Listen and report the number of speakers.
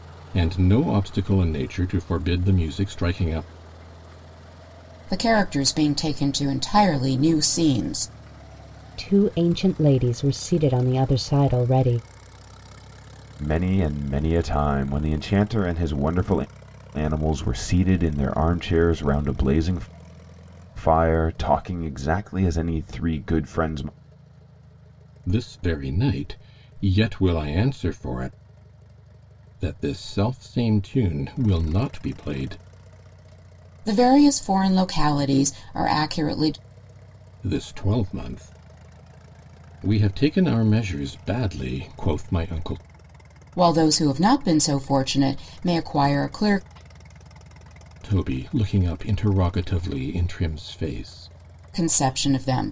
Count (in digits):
4